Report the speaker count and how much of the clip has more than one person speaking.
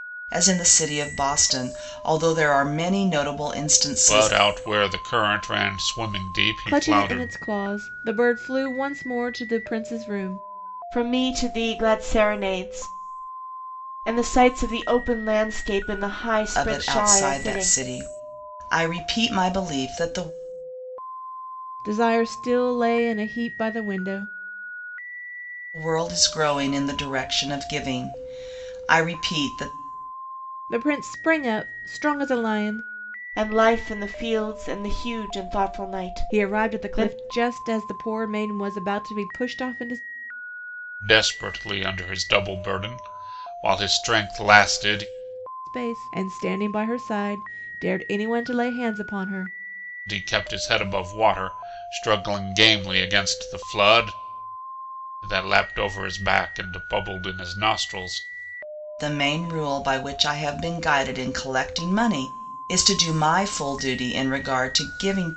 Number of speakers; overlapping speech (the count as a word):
four, about 5%